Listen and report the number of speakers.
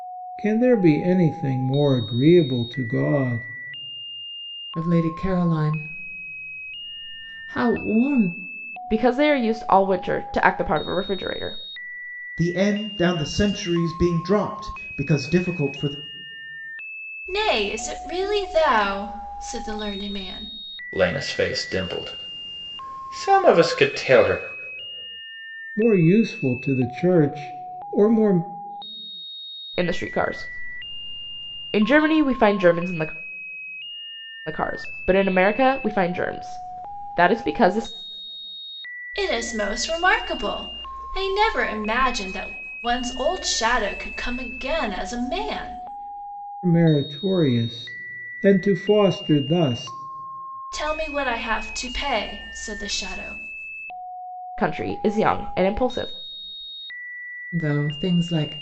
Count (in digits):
6